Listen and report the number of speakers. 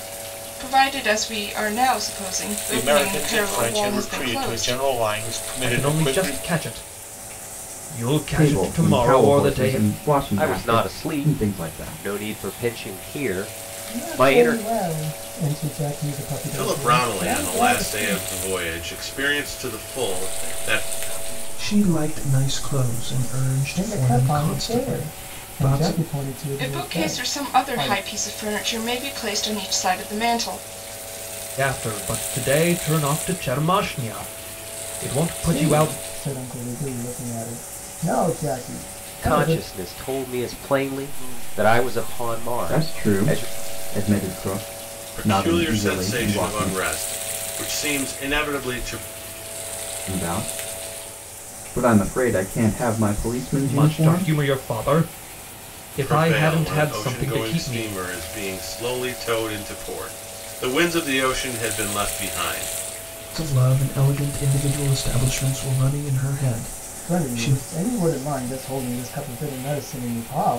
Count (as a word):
nine